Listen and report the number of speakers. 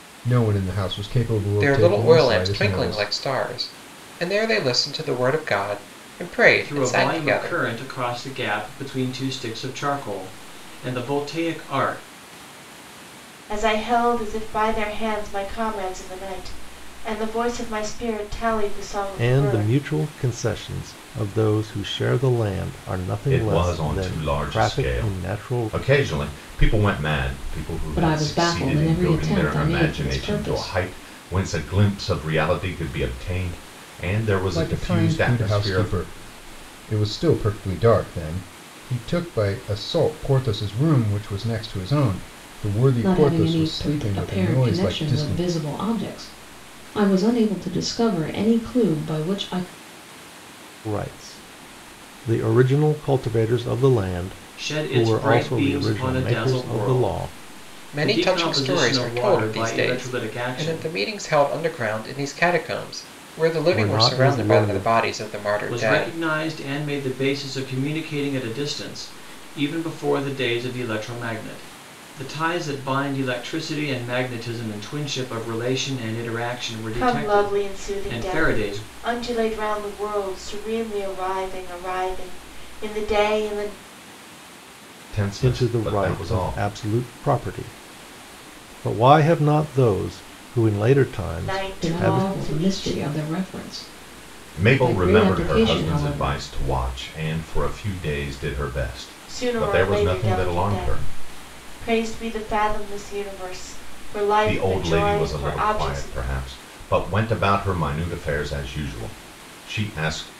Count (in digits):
7